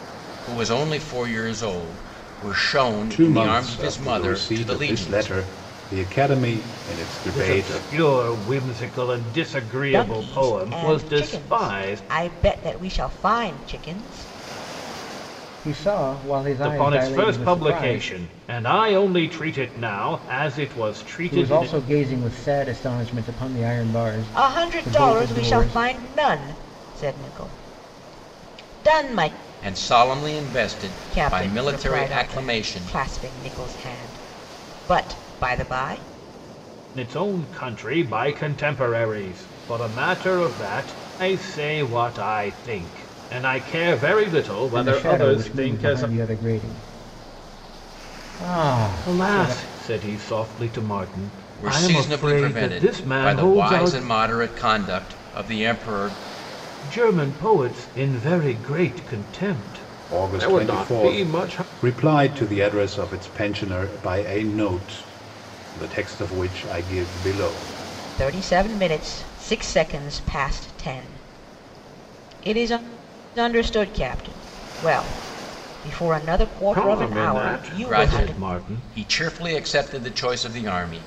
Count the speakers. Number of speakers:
five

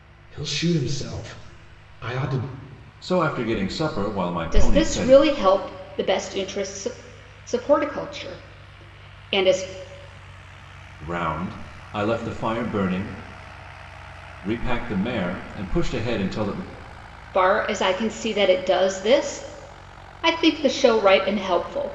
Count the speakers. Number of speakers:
three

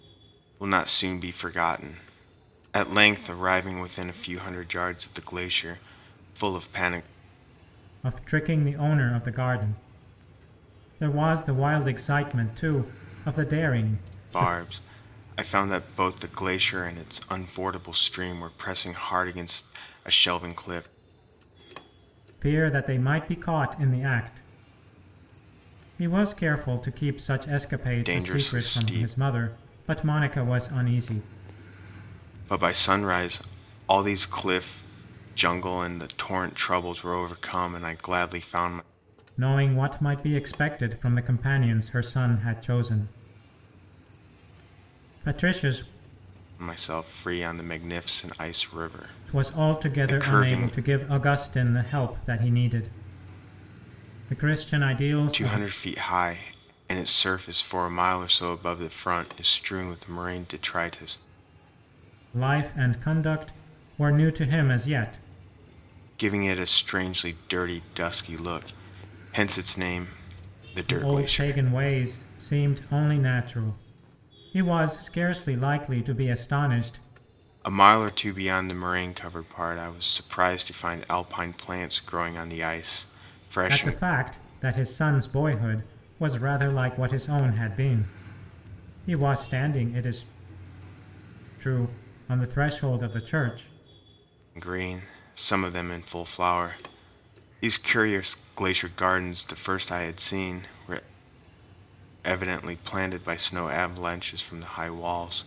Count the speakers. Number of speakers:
two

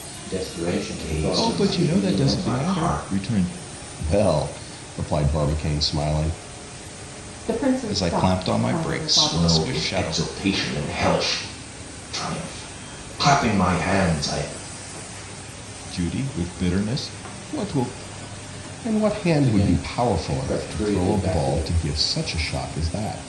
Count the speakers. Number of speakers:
six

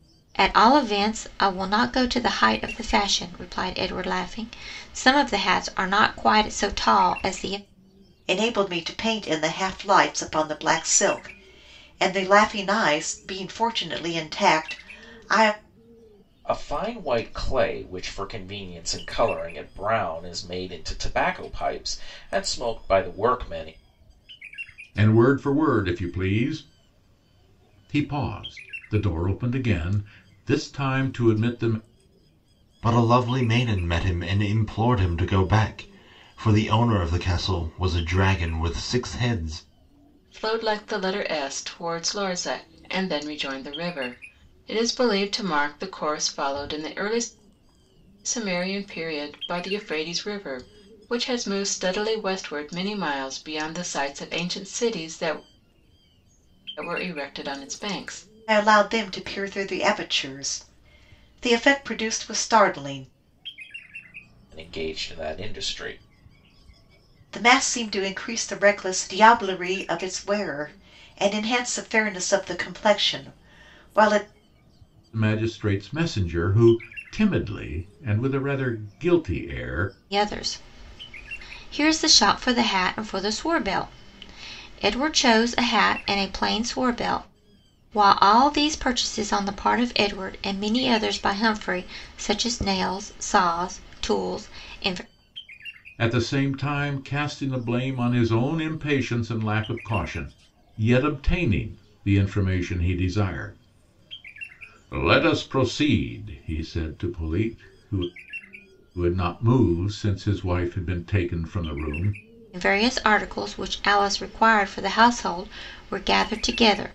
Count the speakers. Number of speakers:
six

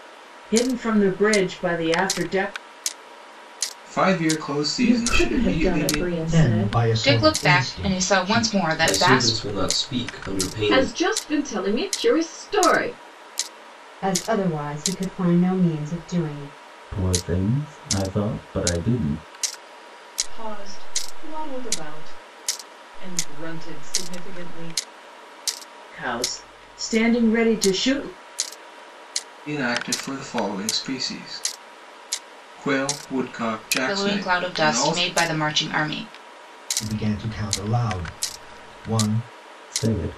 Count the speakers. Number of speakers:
ten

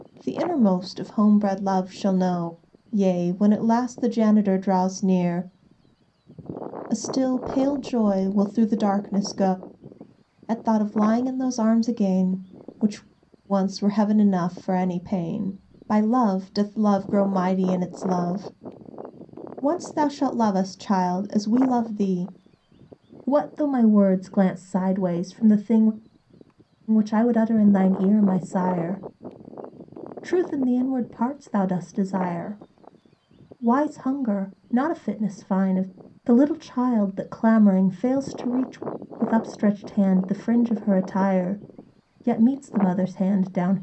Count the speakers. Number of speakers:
one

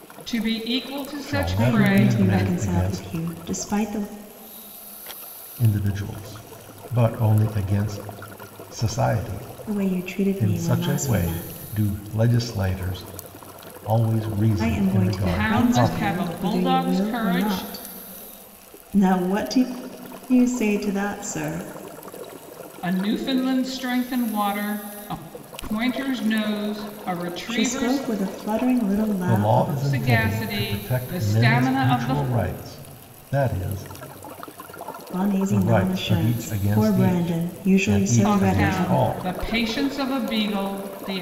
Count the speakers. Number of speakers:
three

